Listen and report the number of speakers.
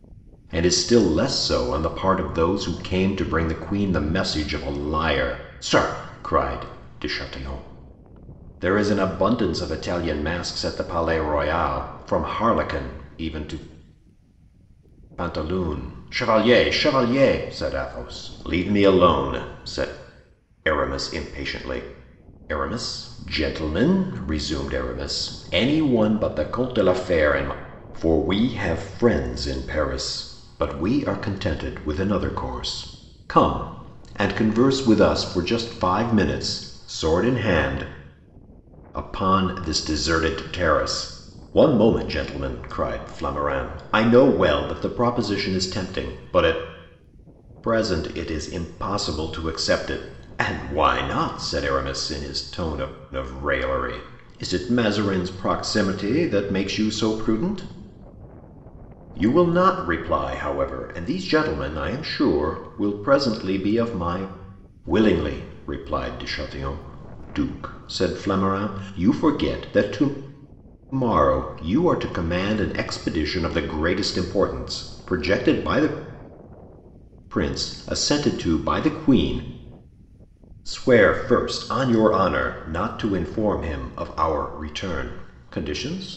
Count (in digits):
1